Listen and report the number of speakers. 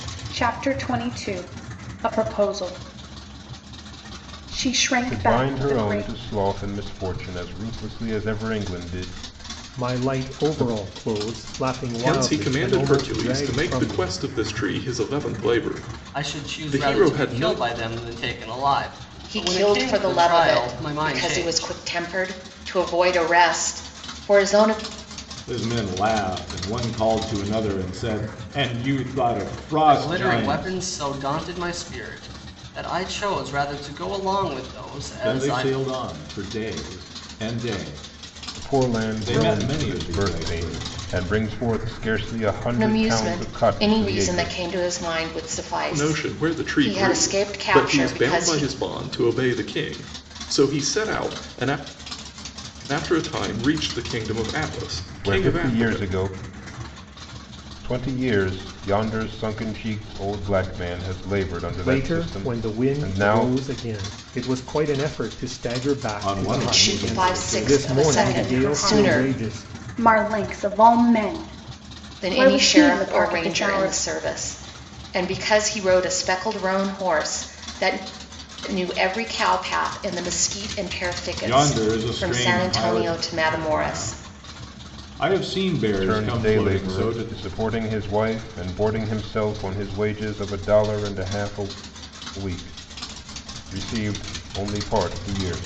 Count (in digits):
7